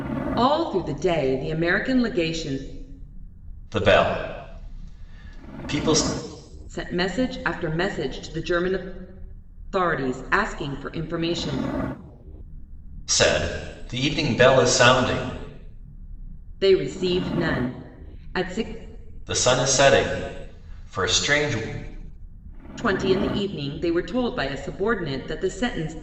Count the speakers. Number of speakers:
2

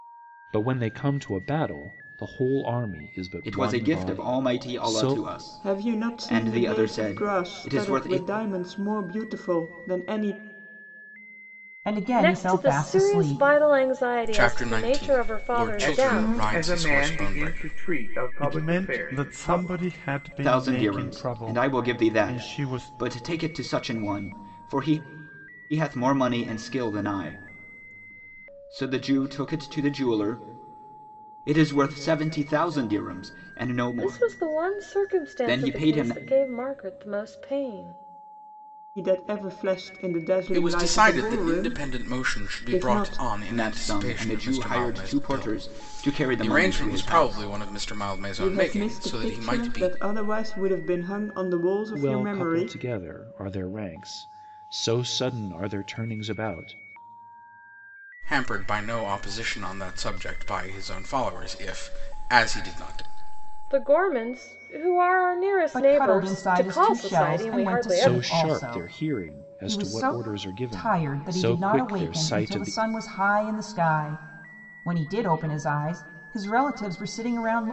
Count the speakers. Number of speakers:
8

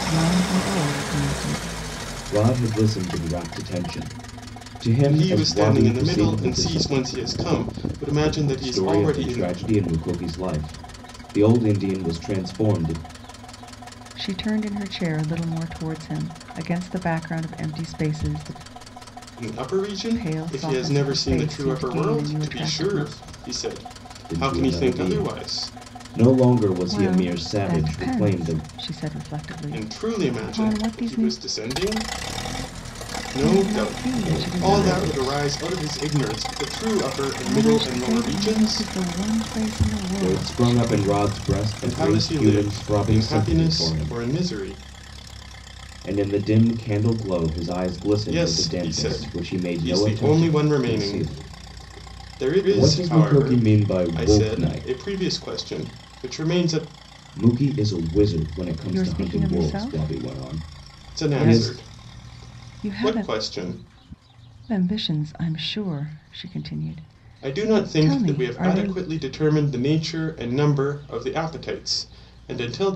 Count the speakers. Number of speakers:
3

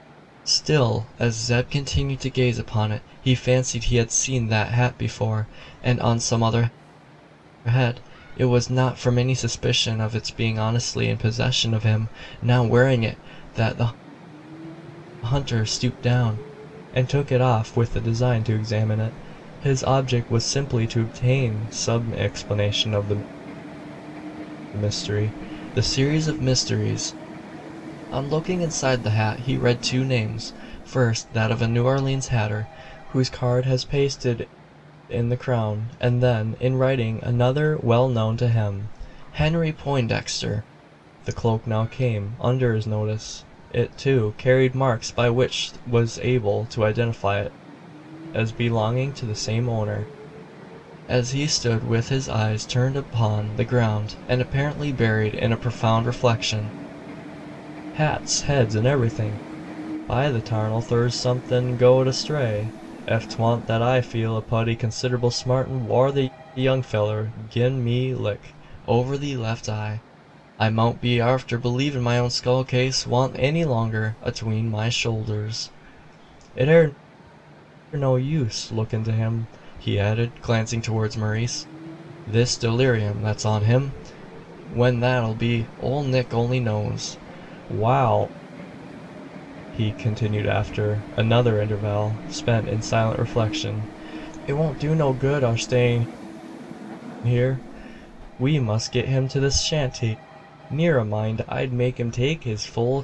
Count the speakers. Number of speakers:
1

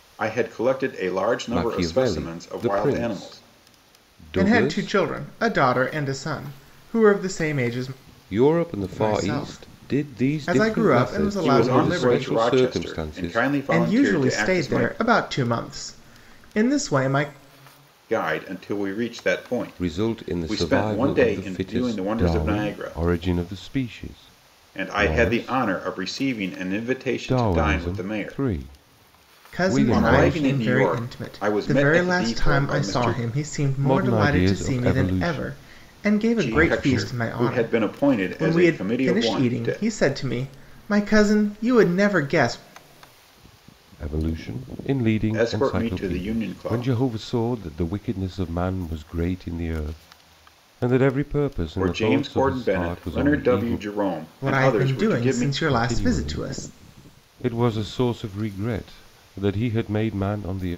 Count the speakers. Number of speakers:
3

